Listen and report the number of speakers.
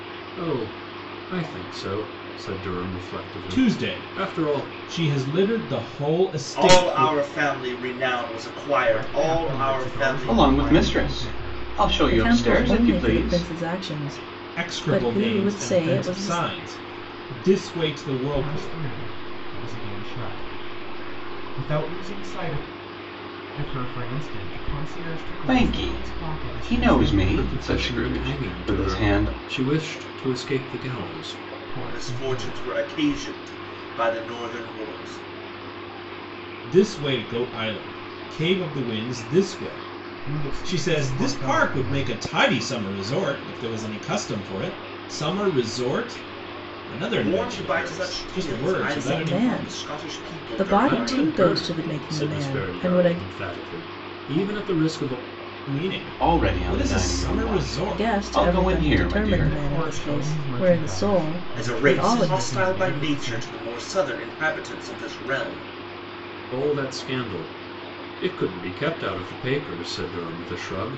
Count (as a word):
six